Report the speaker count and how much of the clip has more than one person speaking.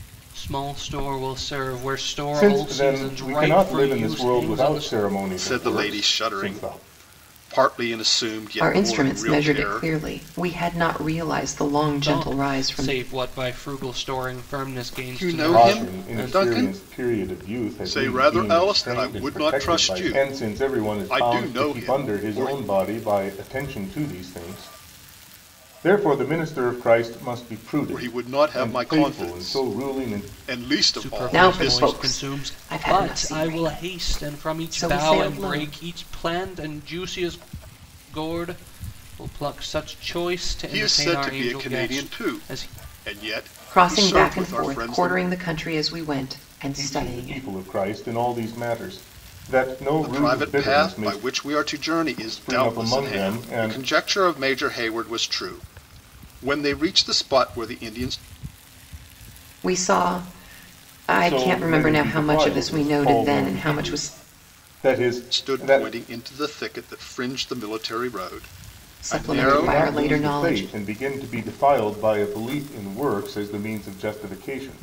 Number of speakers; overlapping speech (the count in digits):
4, about 43%